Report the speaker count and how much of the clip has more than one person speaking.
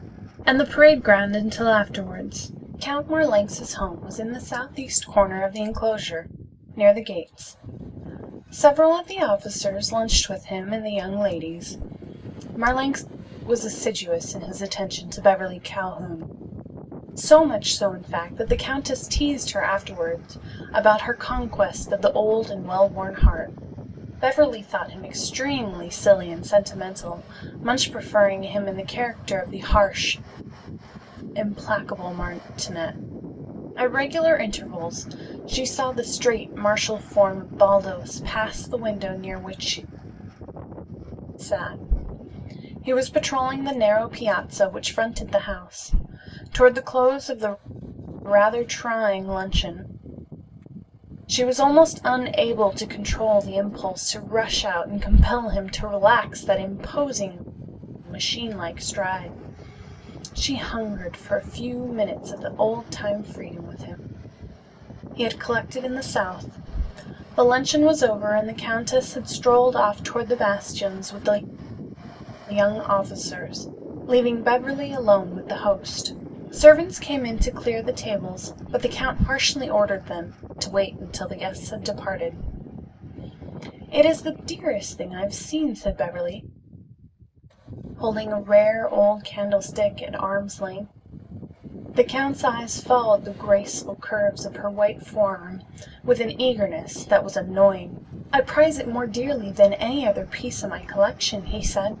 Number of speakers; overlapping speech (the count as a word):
one, no overlap